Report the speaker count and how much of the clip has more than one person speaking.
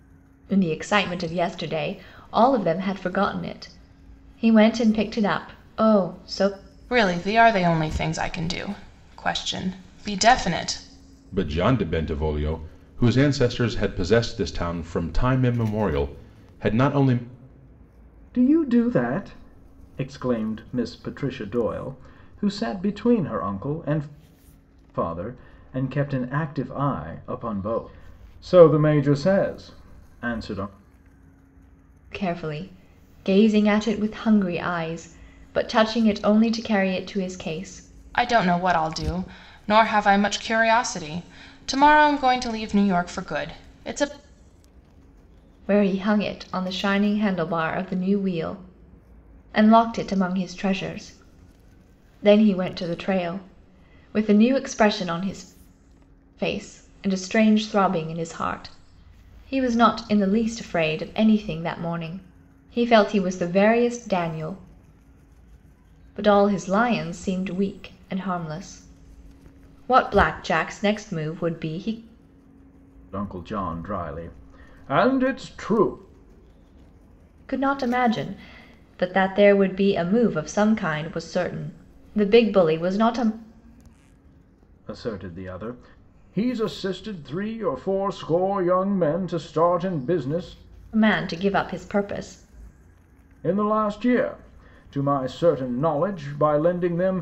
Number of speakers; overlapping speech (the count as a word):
four, no overlap